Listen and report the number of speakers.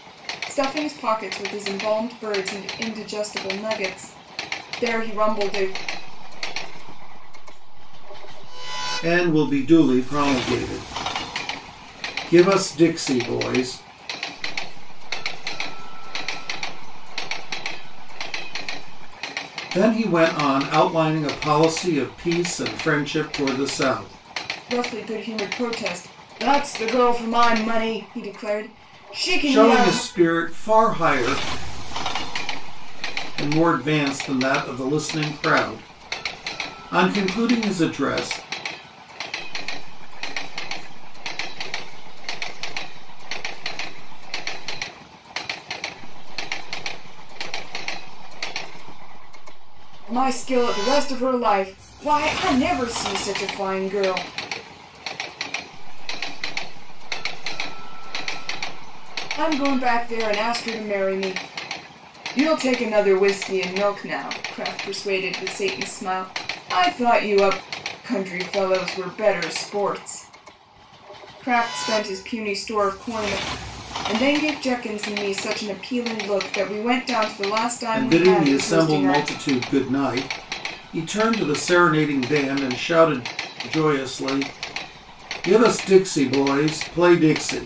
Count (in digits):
3